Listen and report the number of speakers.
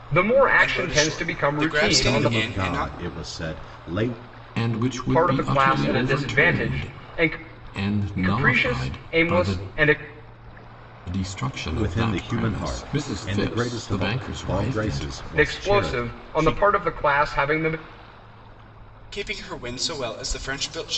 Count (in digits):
4